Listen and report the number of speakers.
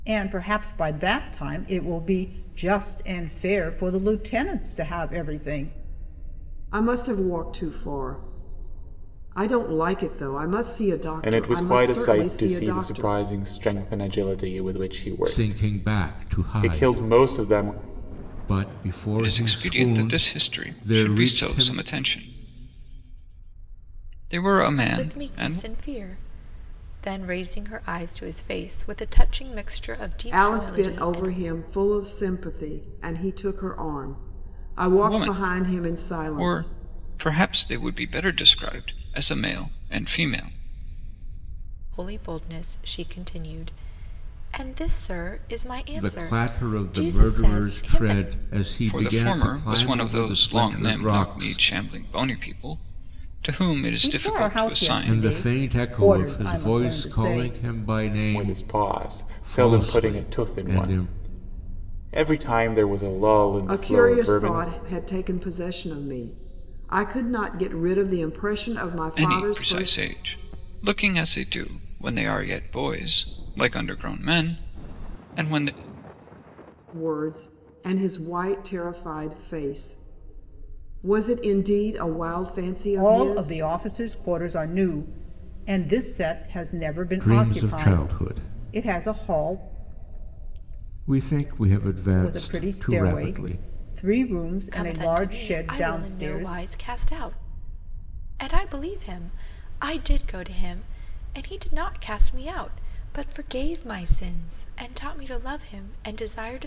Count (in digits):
6